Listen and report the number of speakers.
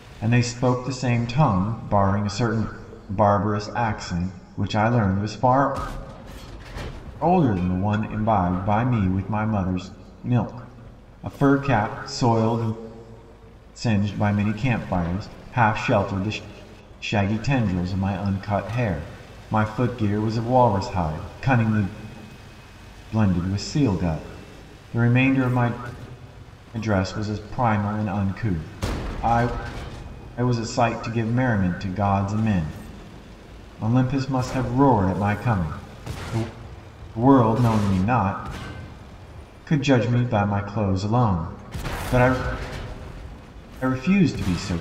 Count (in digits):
1